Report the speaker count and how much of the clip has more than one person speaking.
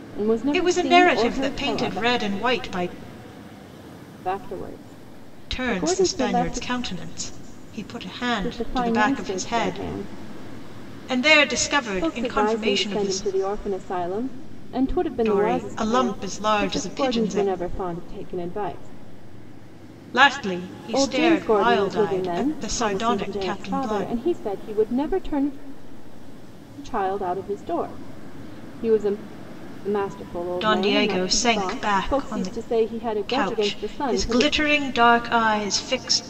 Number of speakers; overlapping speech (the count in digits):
2, about 40%